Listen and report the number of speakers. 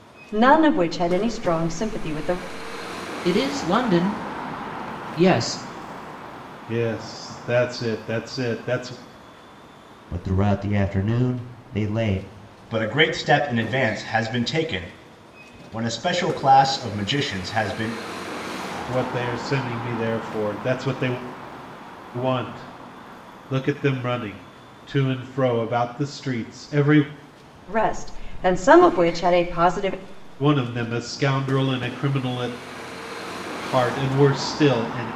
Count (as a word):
five